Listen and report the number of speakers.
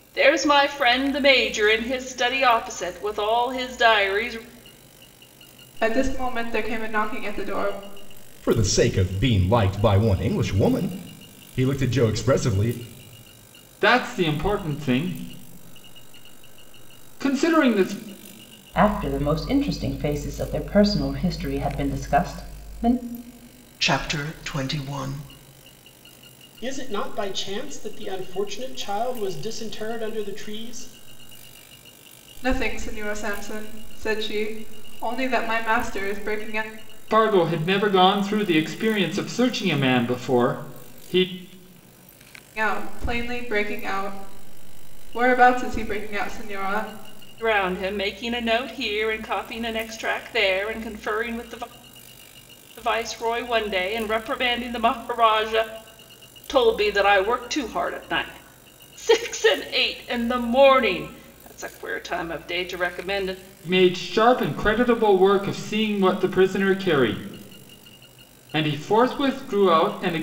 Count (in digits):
7